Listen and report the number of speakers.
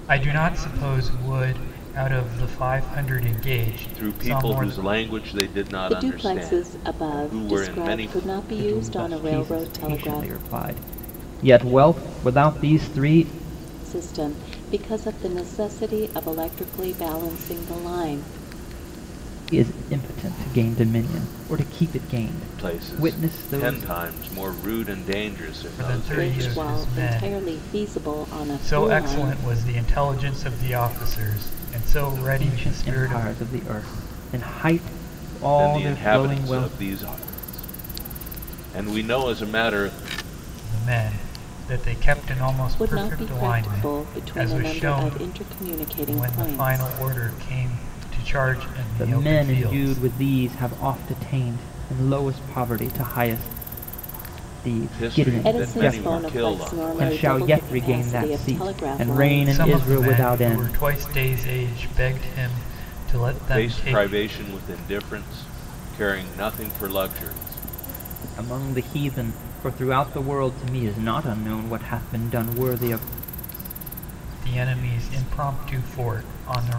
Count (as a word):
four